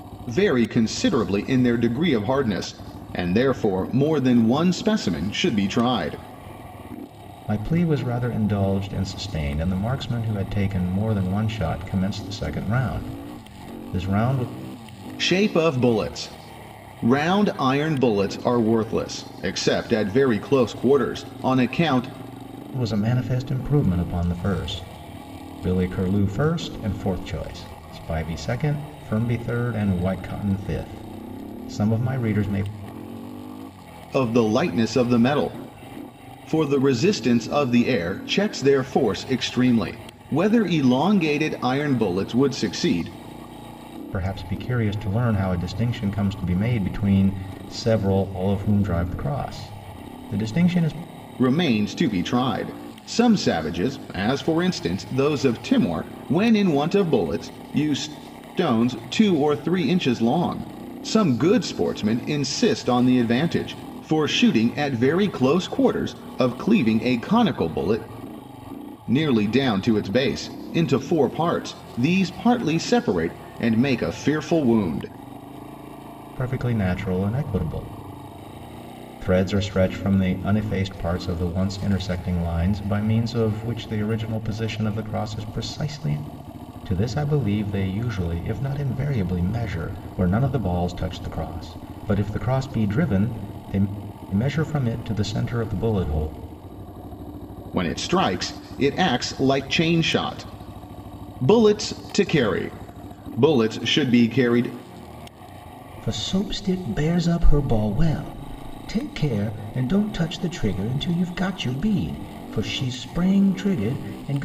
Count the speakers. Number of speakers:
two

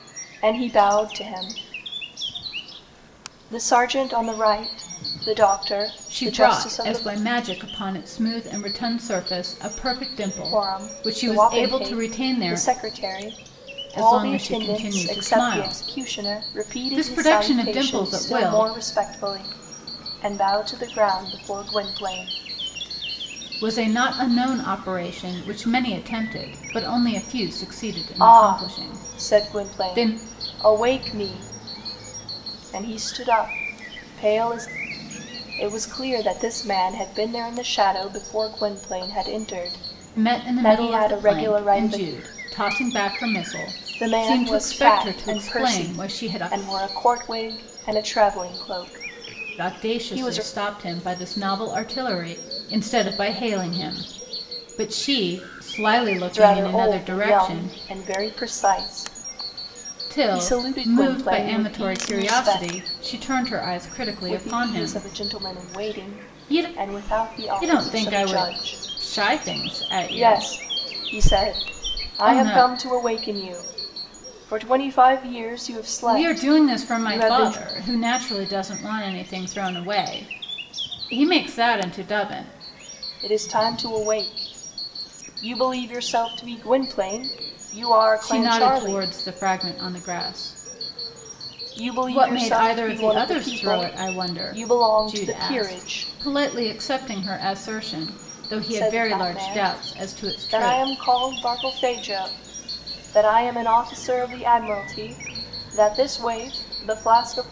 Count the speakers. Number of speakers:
two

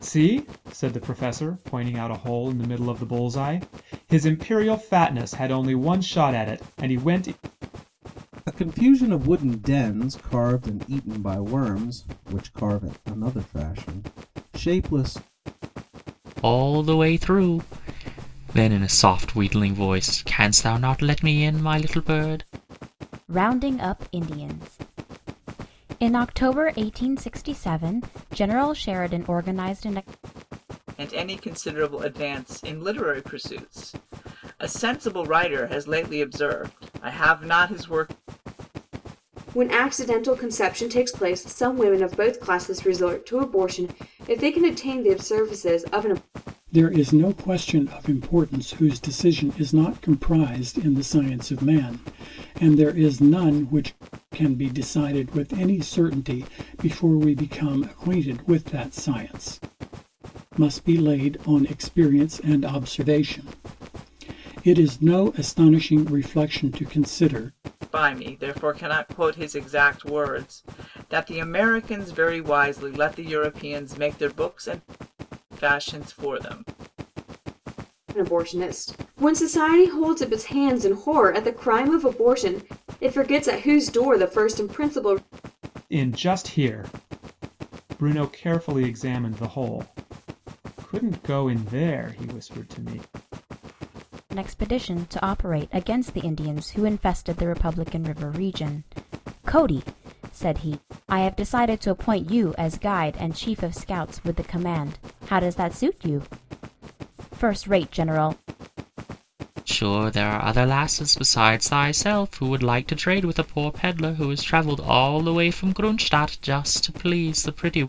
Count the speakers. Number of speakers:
seven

